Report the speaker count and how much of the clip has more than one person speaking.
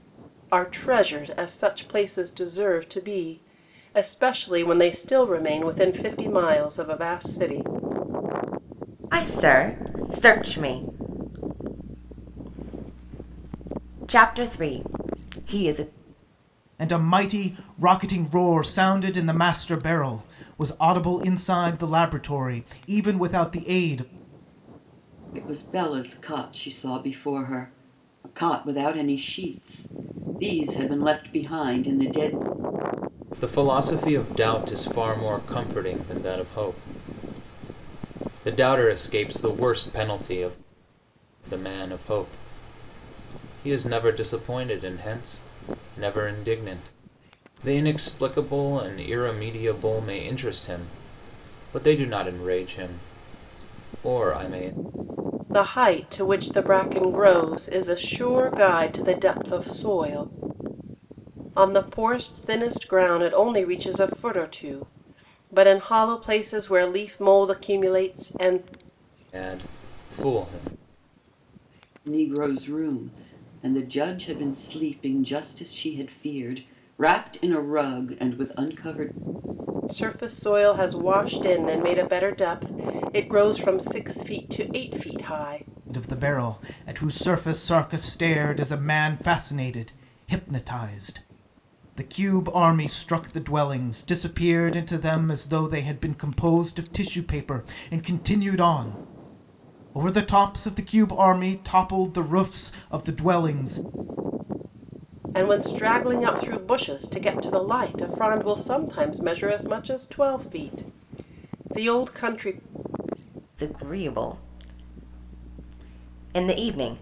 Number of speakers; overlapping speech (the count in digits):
5, no overlap